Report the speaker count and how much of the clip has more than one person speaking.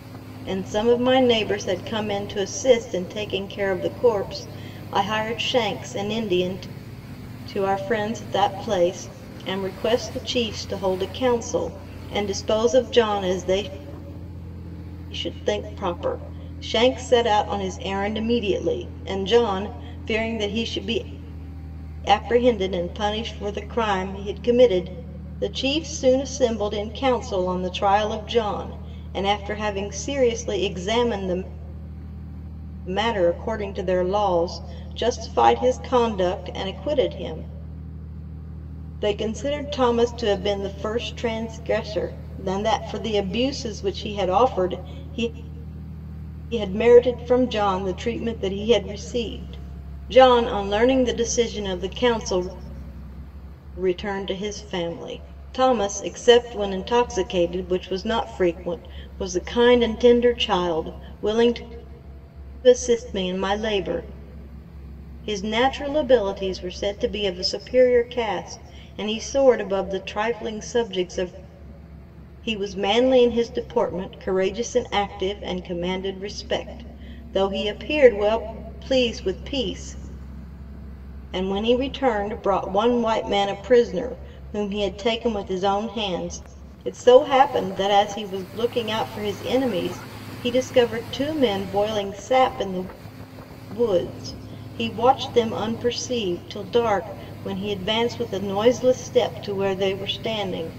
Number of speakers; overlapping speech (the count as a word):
one, no overlap